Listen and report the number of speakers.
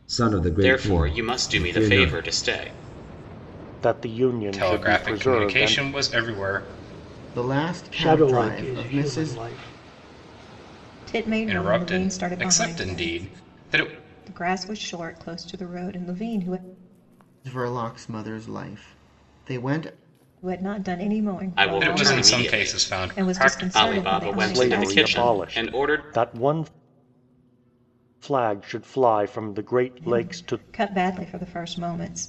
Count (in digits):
7